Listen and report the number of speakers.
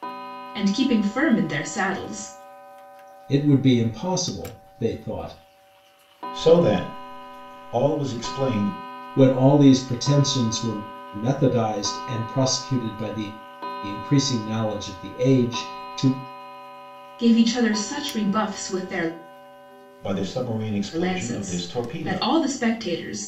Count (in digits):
3